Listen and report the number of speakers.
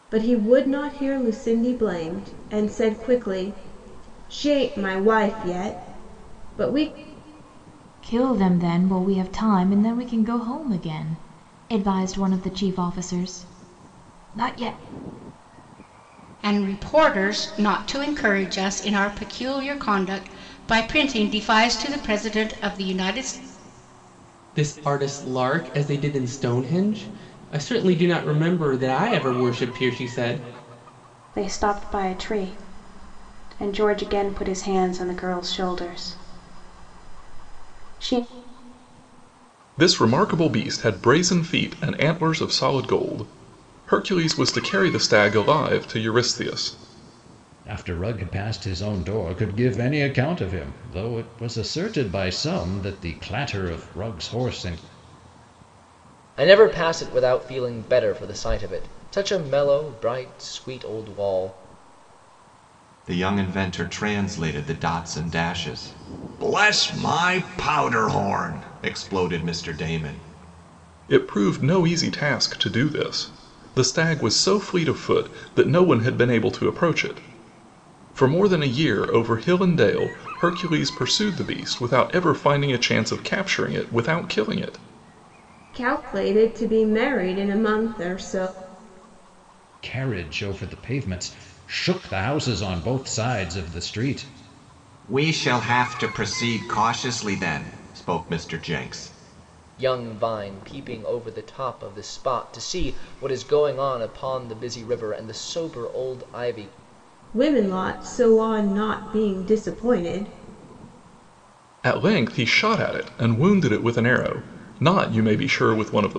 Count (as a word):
nine